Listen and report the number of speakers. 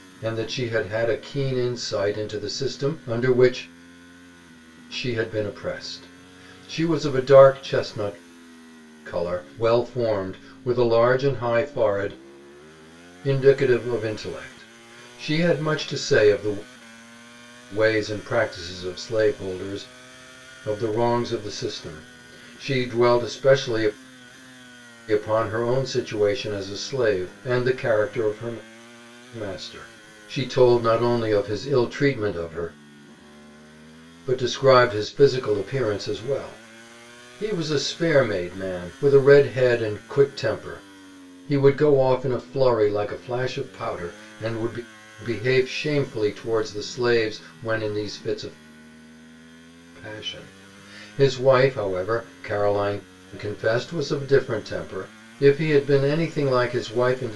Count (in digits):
1